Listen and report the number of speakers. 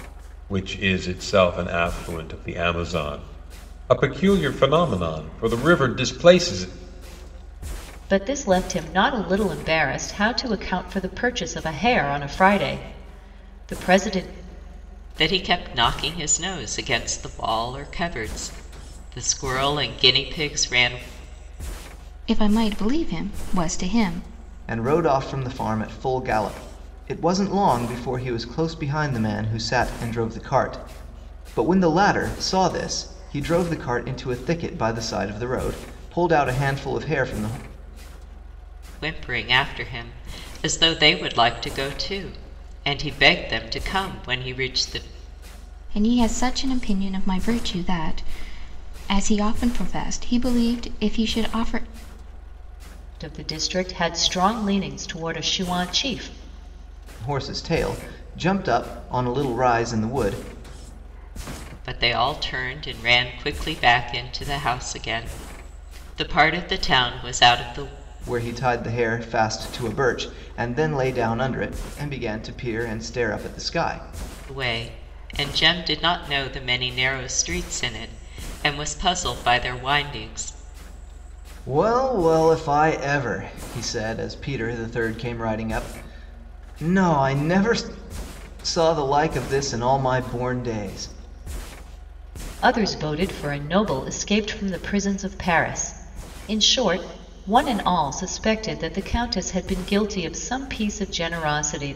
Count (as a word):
five